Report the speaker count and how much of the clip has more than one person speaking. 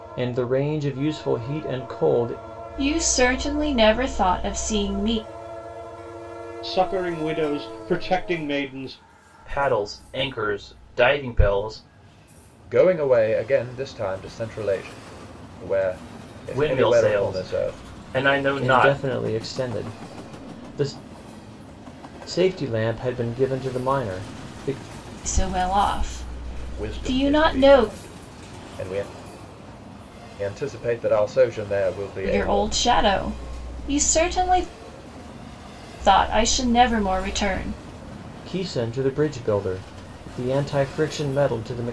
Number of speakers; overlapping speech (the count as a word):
five, about 8%